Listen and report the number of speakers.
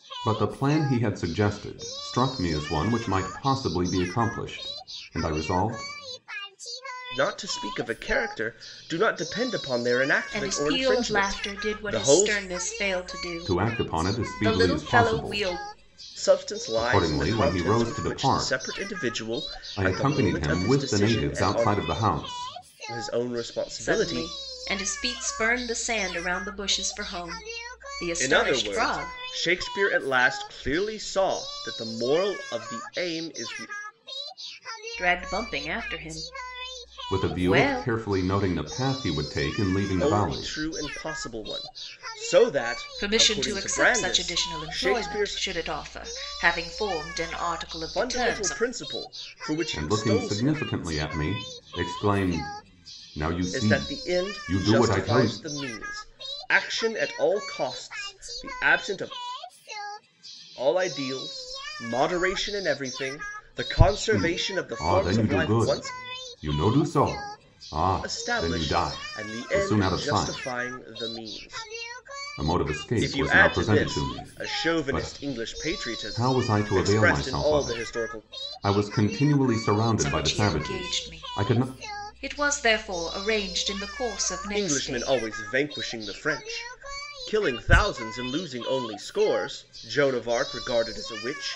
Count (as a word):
three